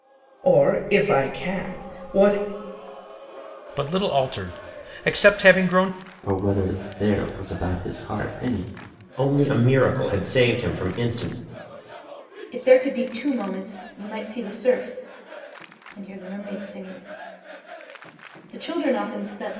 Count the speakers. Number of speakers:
5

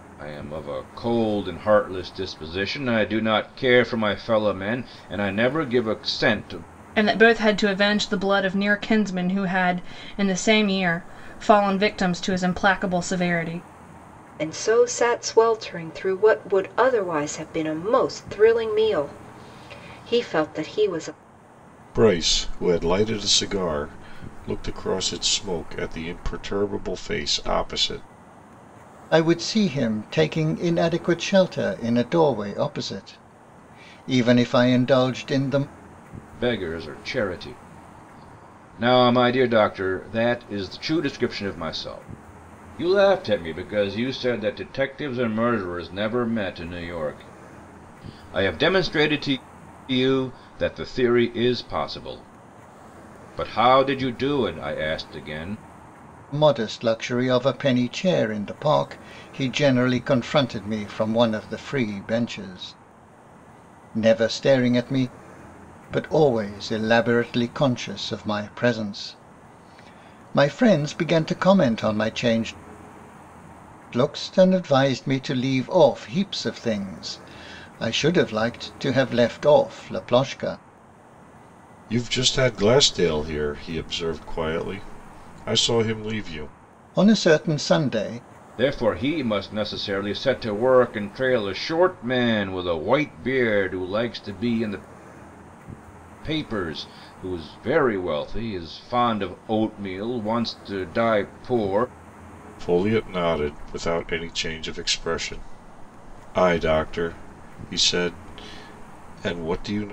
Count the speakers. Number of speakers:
5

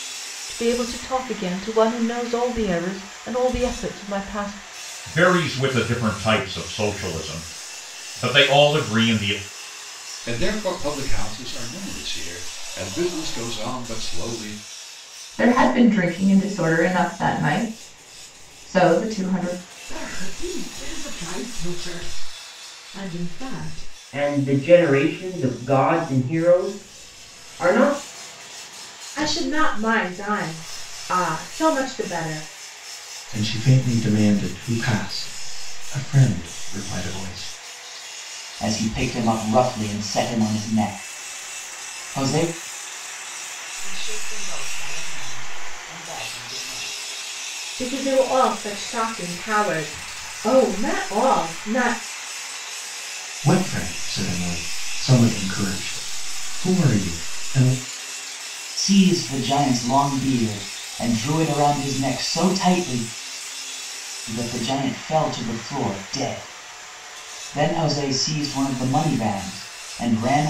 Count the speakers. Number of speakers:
10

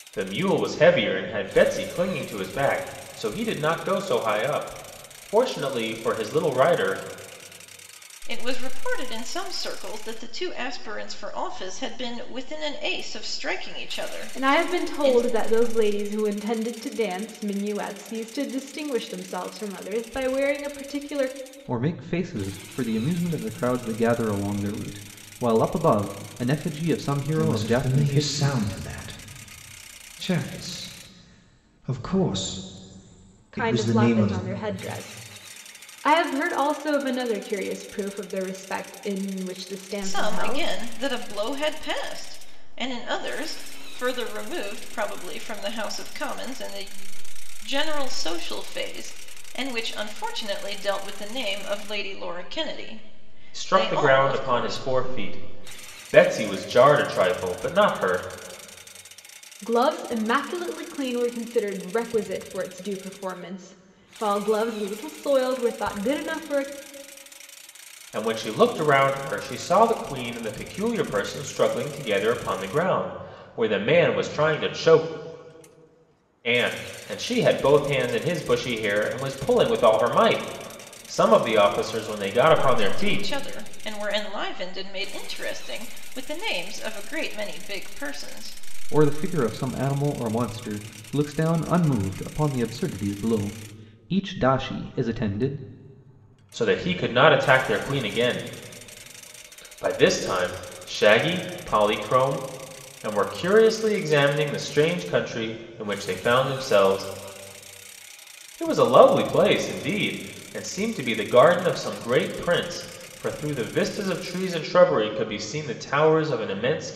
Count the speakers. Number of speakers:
5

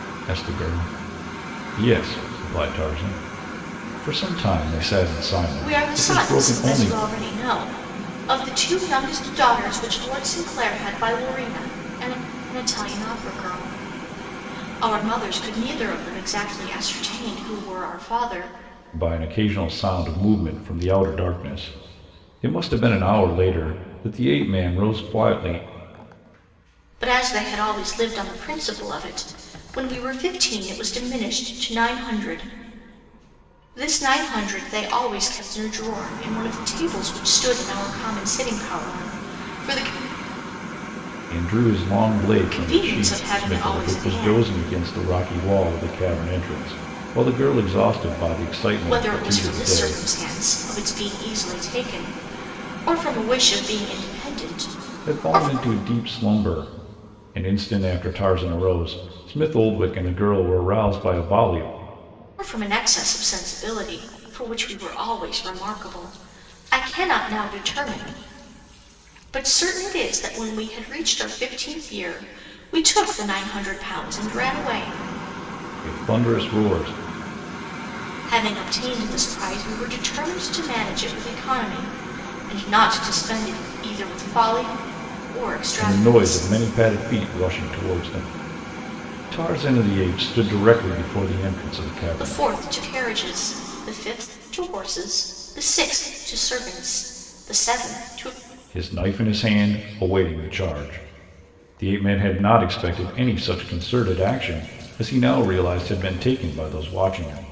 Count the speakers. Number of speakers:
2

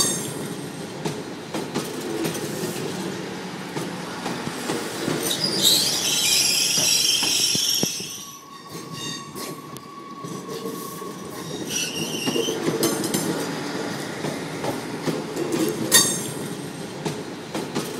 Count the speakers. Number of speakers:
0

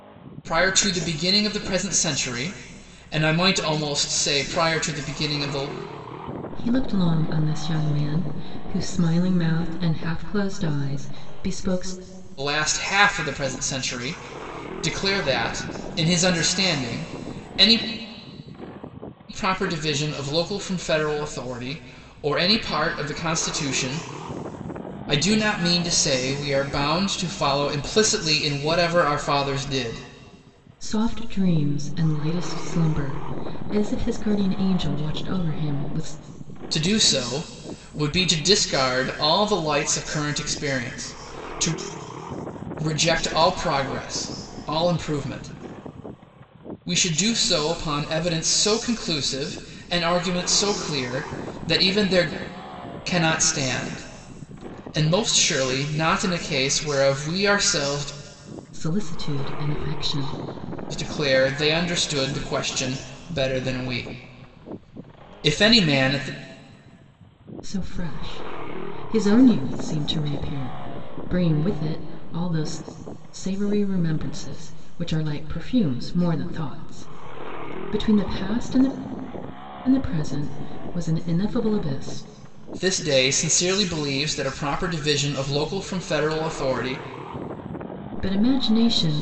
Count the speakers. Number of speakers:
2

